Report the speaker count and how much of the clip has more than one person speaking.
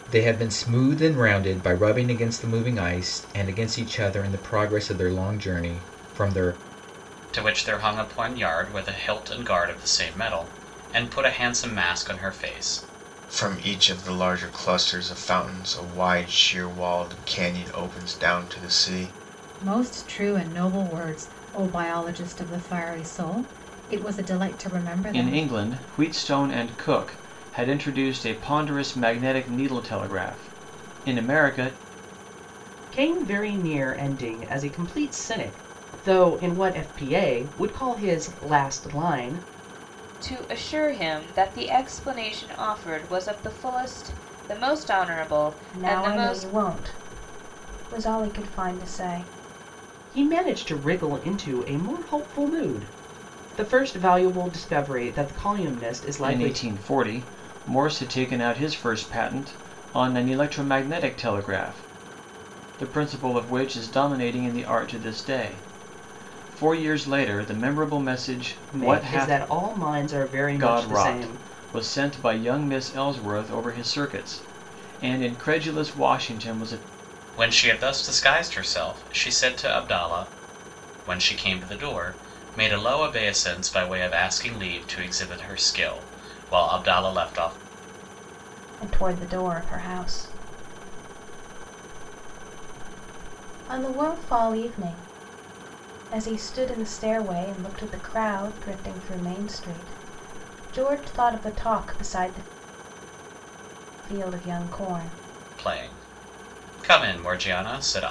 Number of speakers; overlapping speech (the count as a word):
eight, about 4%